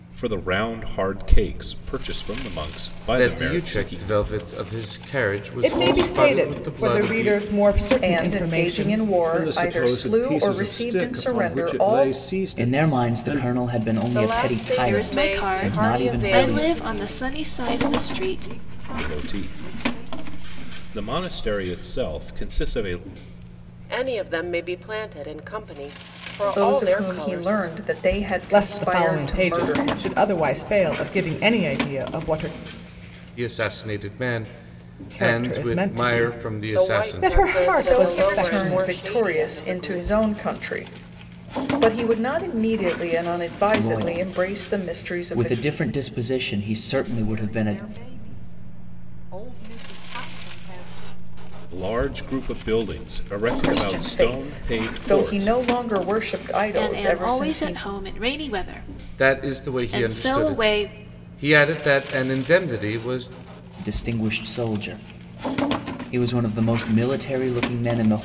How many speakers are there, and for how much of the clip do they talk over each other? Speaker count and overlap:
9, about 42%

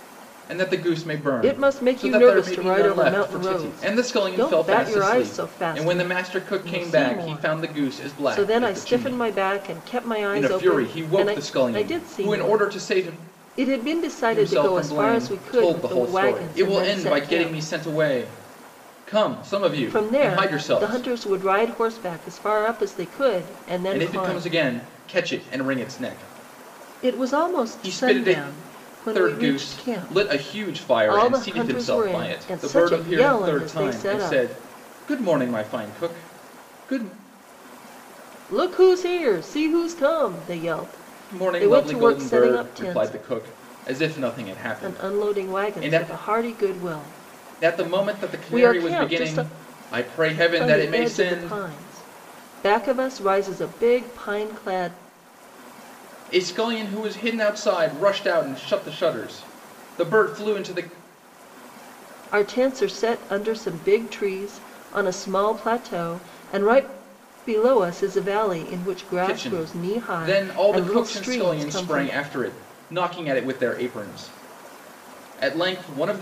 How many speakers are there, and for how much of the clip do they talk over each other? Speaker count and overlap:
2, about 42%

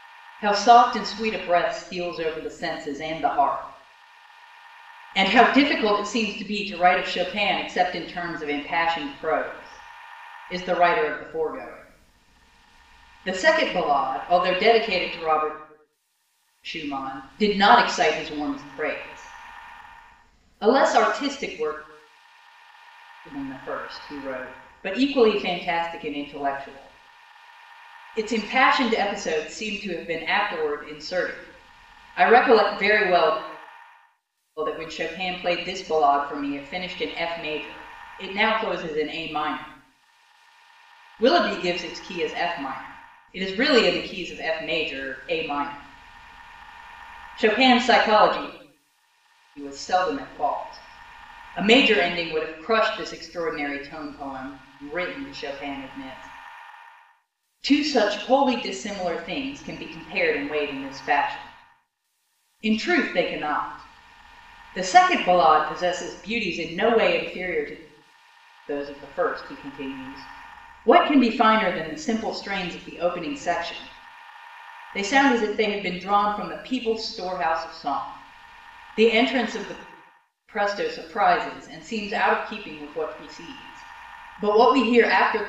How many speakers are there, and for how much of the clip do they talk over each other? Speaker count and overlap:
1, no overlap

